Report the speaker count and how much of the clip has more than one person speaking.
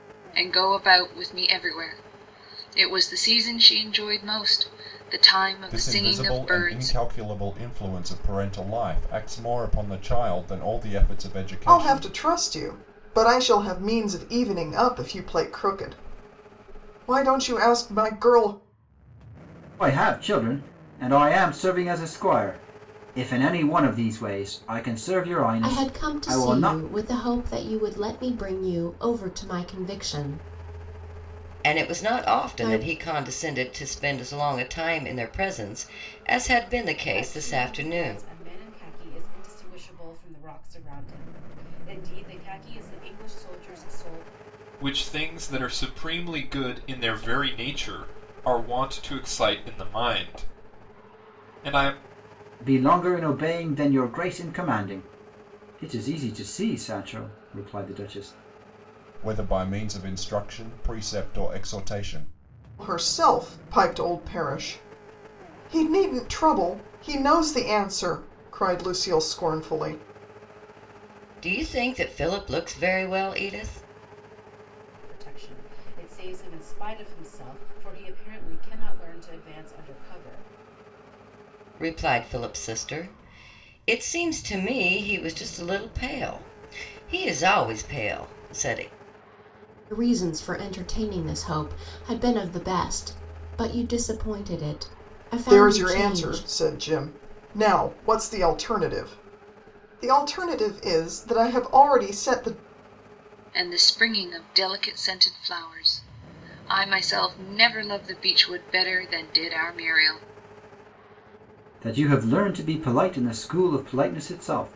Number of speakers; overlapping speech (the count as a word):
eight, about 6%